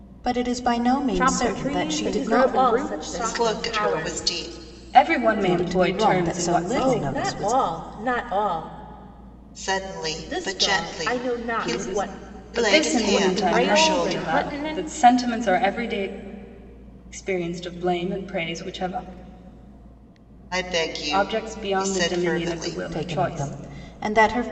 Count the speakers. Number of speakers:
five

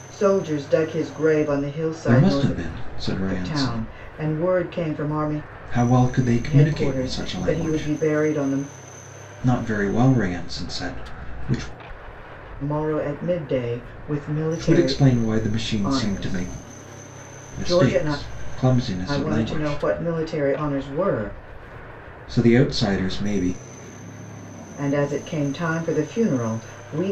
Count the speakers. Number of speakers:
two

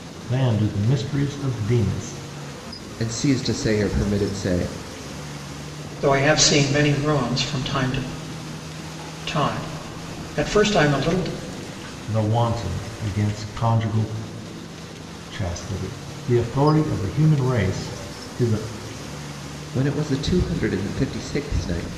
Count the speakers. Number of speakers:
three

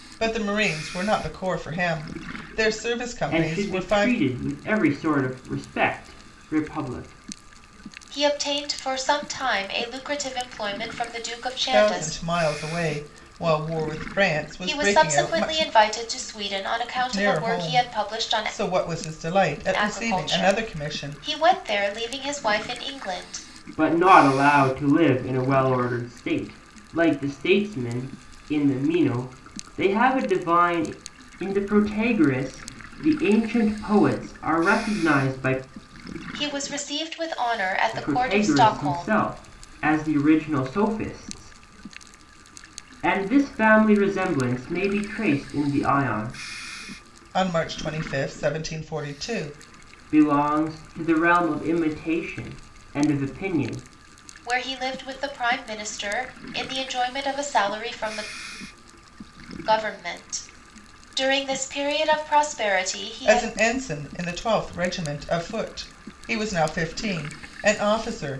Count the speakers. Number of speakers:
three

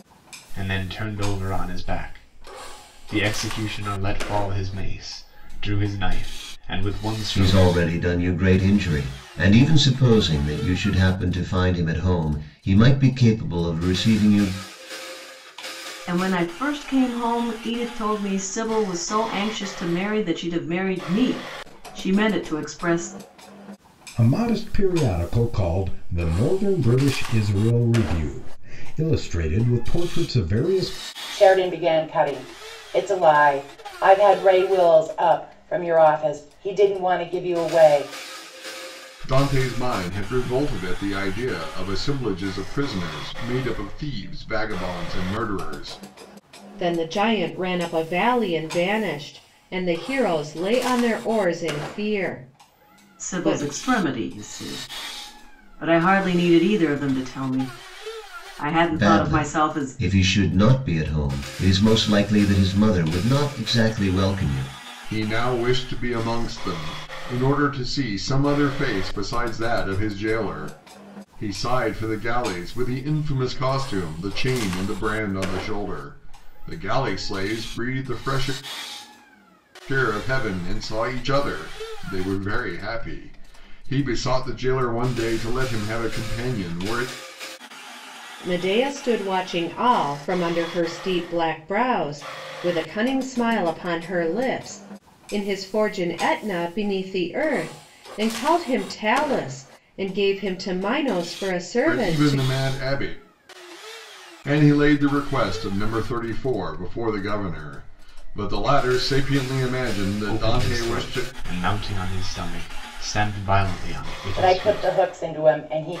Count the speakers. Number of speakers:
seven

